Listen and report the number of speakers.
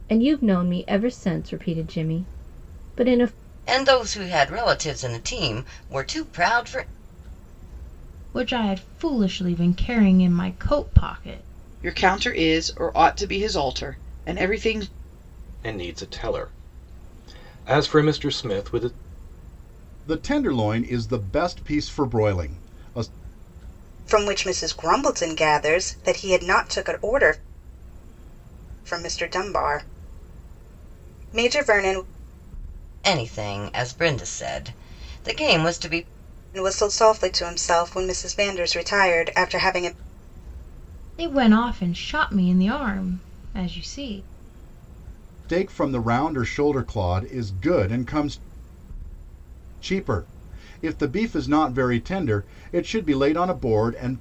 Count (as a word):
seven